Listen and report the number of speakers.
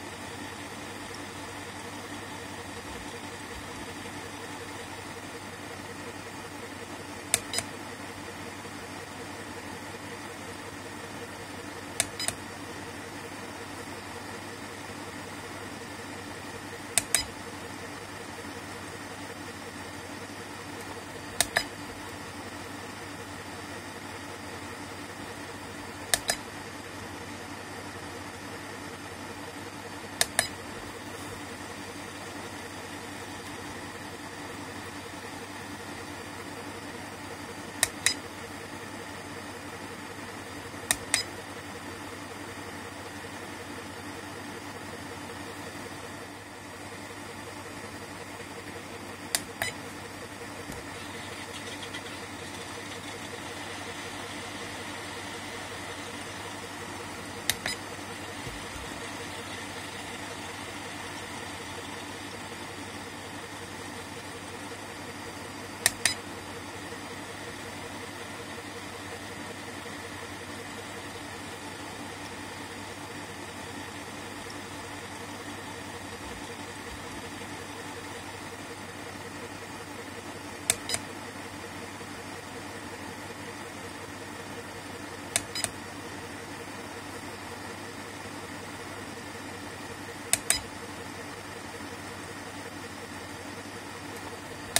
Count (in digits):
0